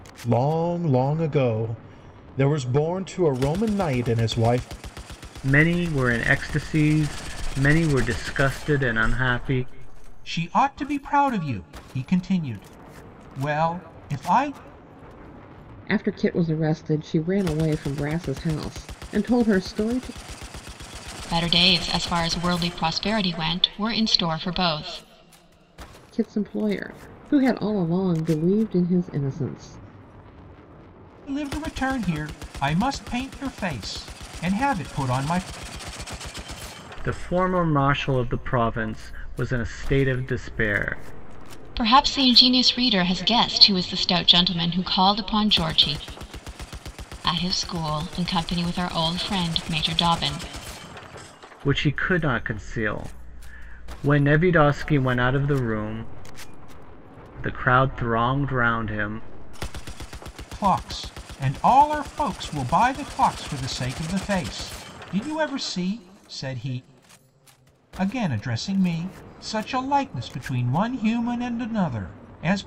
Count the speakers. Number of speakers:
5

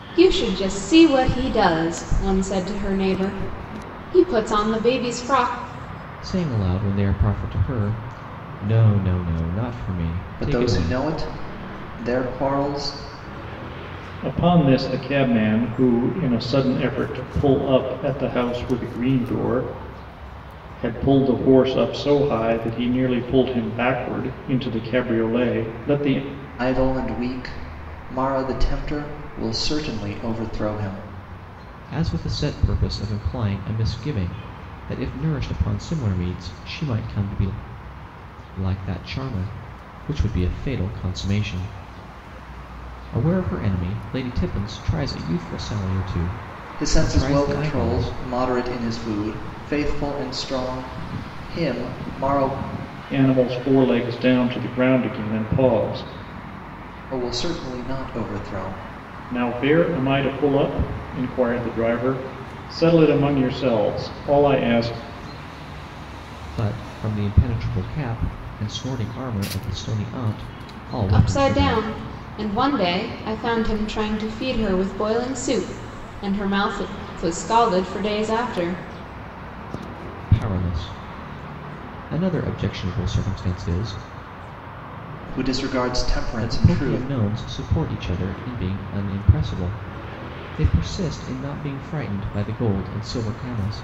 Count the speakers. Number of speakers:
4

